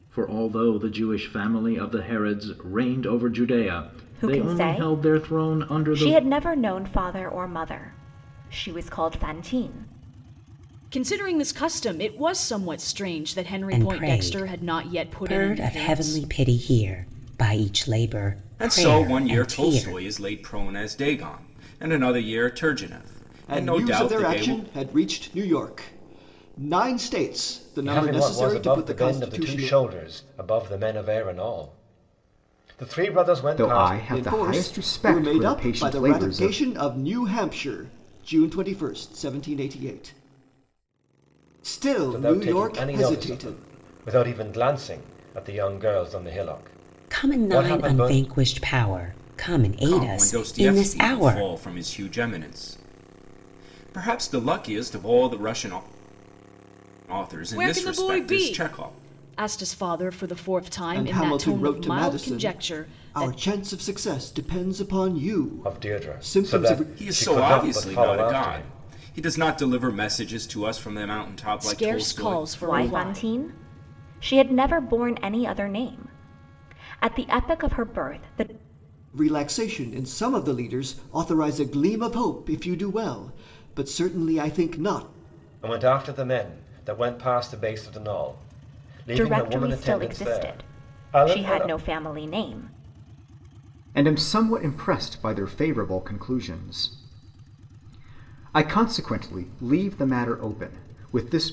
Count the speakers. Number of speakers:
eight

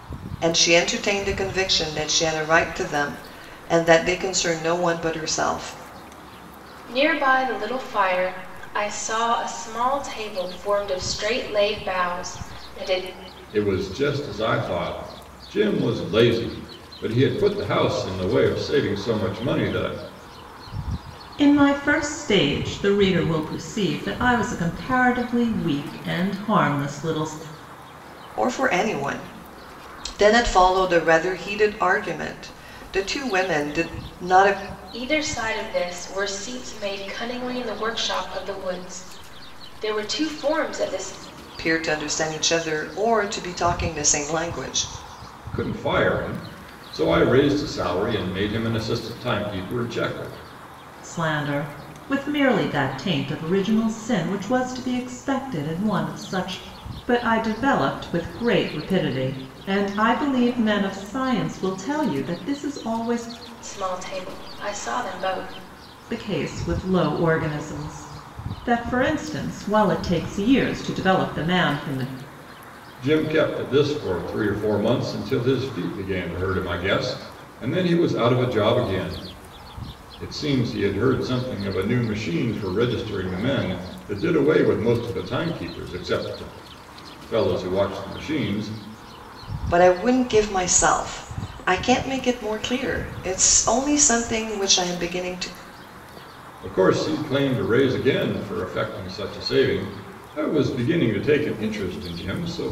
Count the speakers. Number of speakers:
four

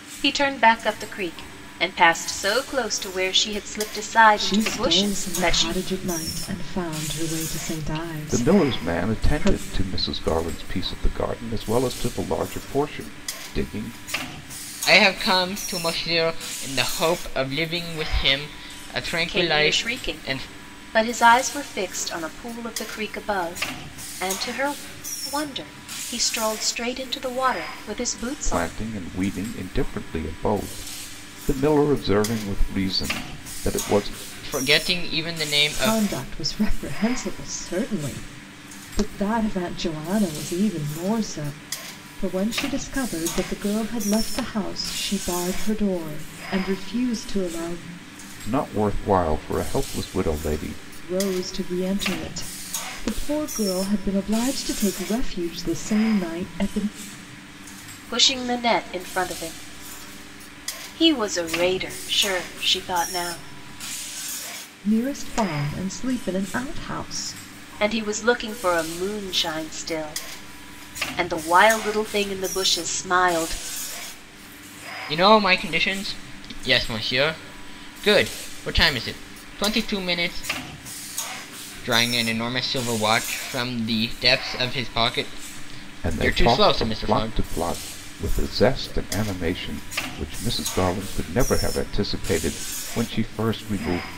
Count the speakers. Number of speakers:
four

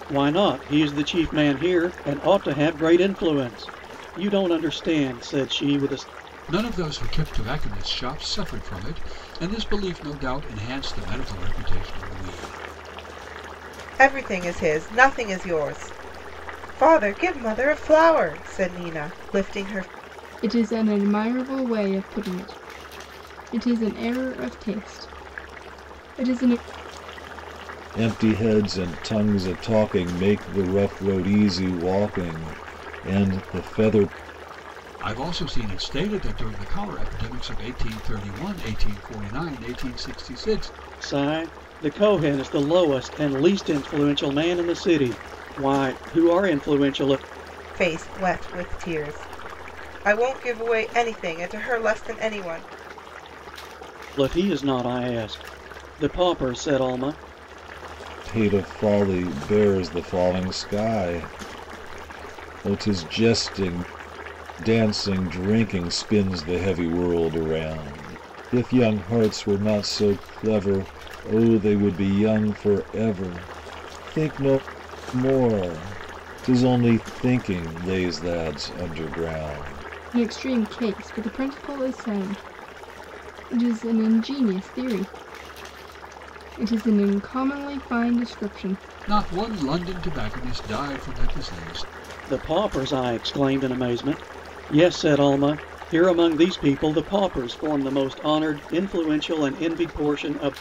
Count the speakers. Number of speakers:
five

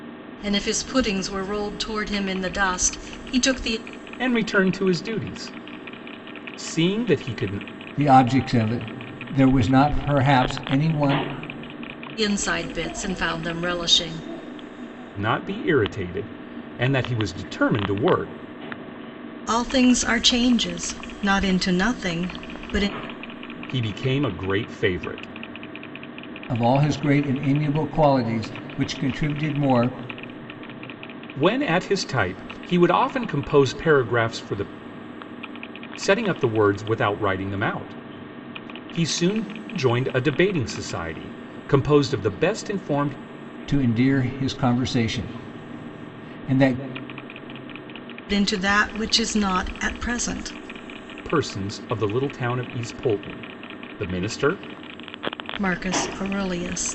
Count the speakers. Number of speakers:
three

